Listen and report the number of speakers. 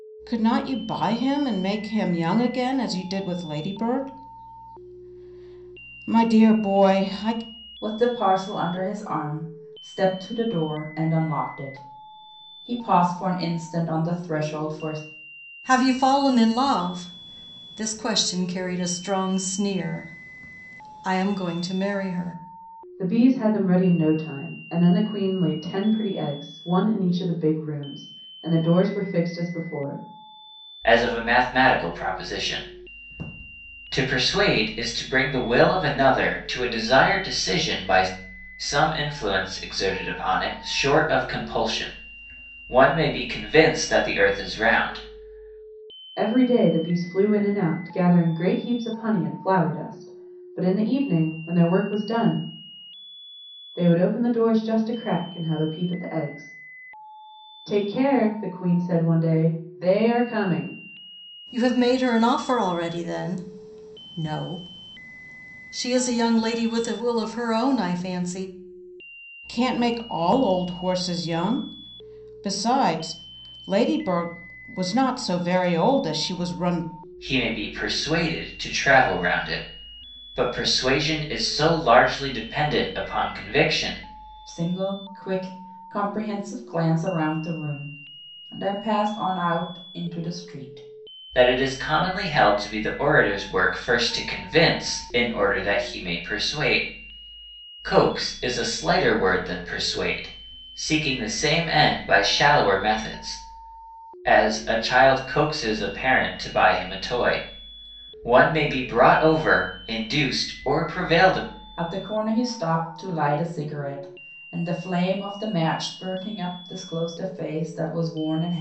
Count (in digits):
5